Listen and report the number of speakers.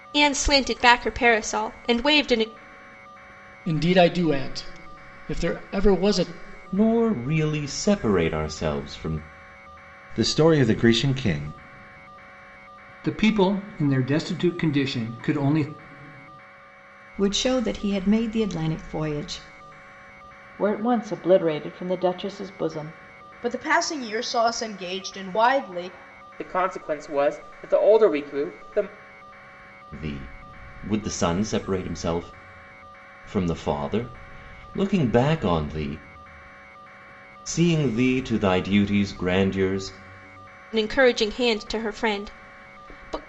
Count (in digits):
9